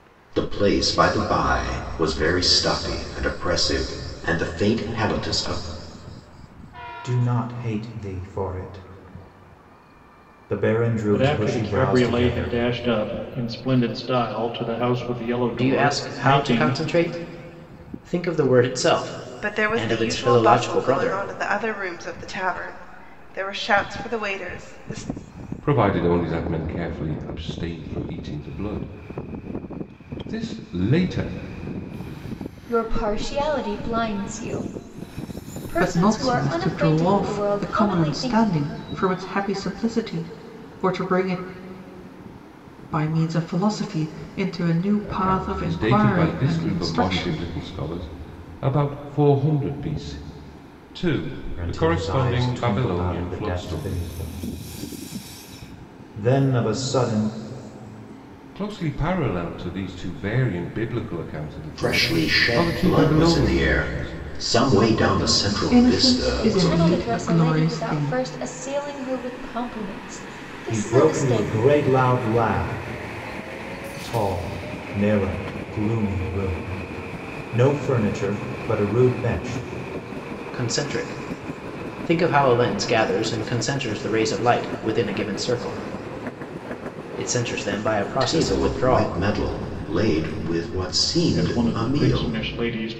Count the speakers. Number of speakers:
8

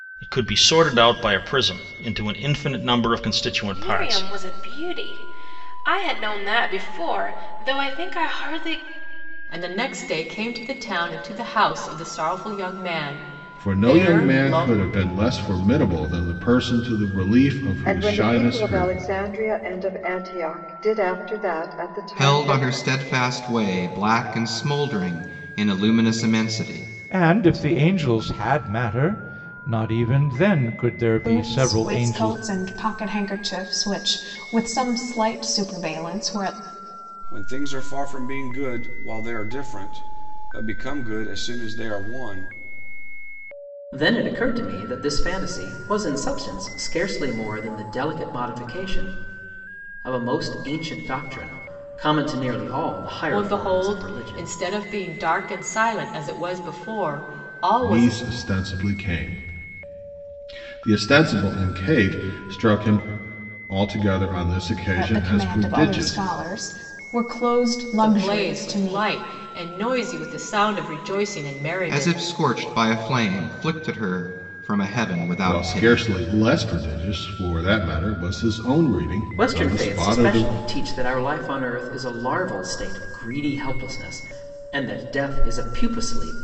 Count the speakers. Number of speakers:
10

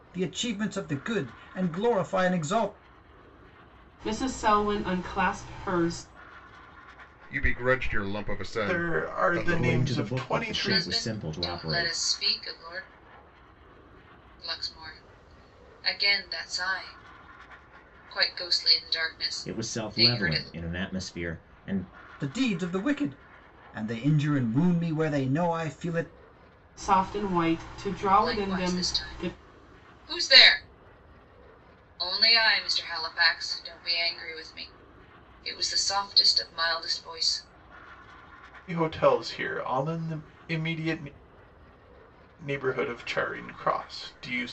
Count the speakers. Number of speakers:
6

